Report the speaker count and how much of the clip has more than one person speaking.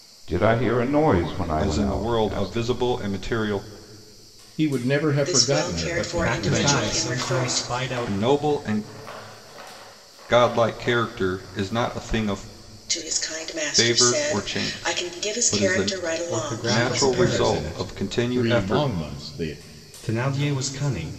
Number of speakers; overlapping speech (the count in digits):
5, about 43%